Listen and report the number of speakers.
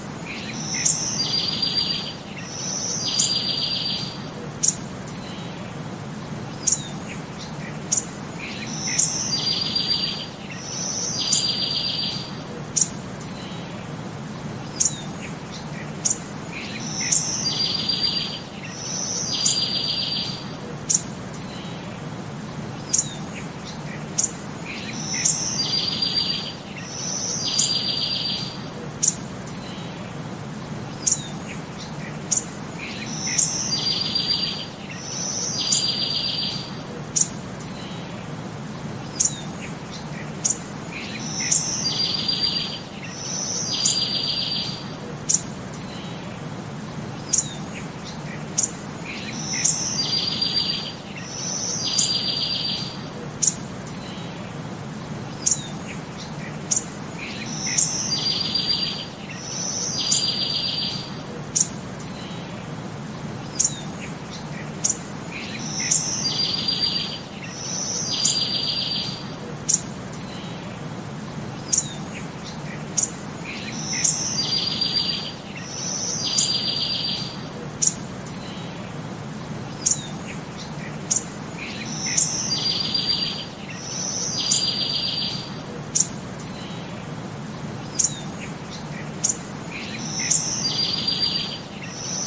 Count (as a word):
zero